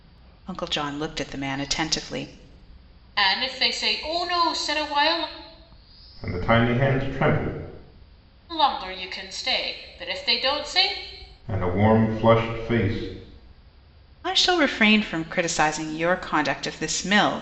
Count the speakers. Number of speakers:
3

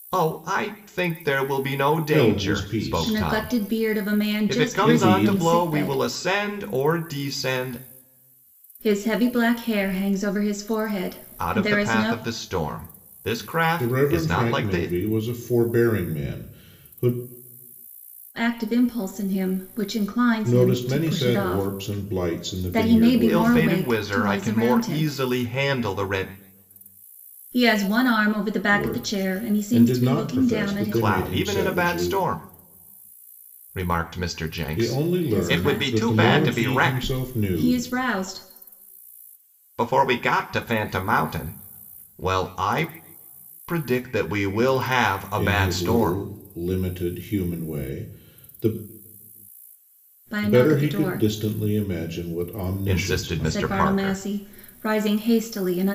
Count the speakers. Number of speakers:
3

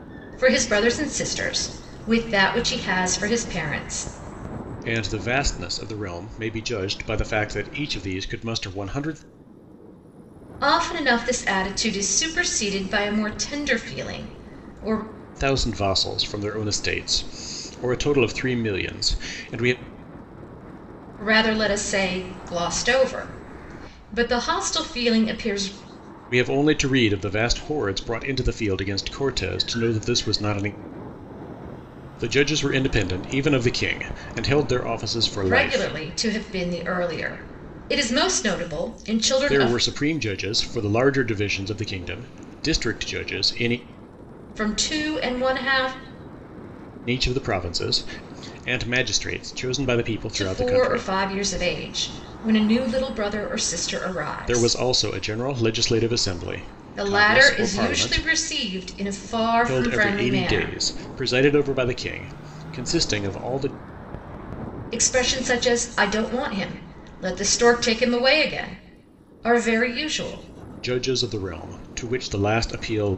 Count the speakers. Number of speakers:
2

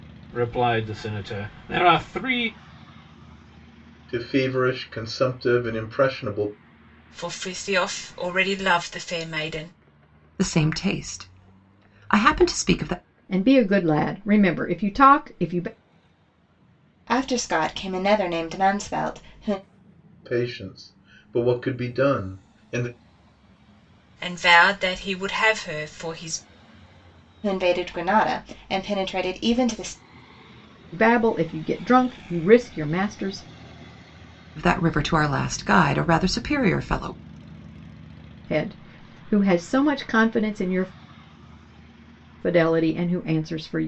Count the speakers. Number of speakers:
6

